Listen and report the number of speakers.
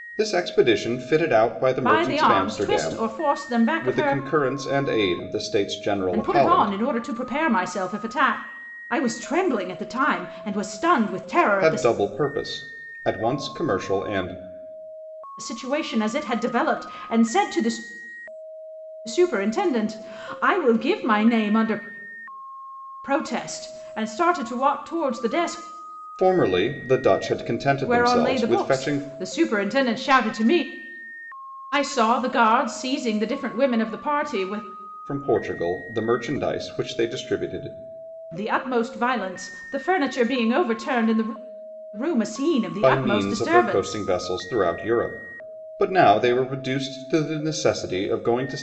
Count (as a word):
two